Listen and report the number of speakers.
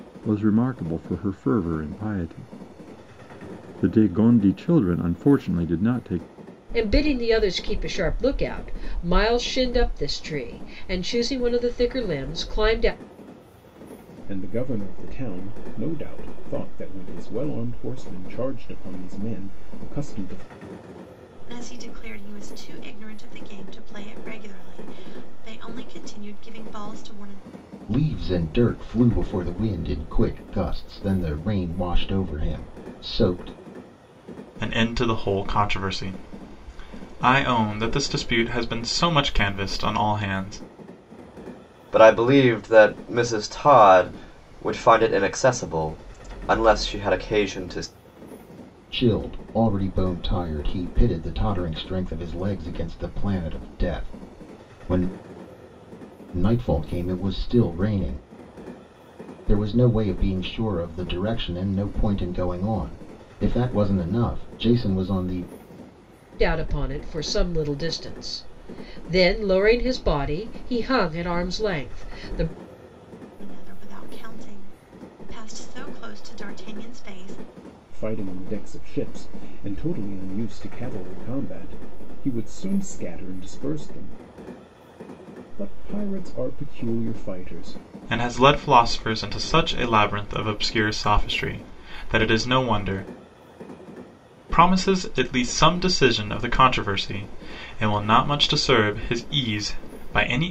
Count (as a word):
seven